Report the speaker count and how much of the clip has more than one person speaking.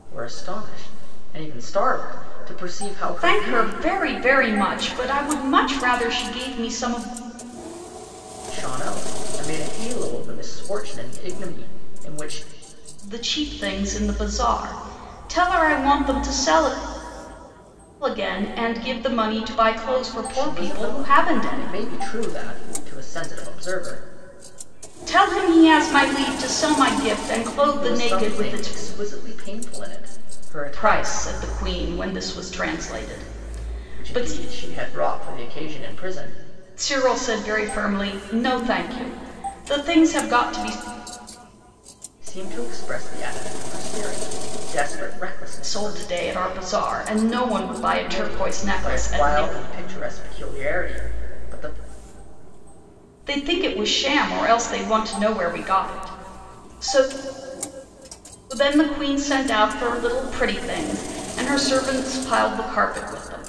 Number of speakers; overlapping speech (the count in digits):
2, about 9%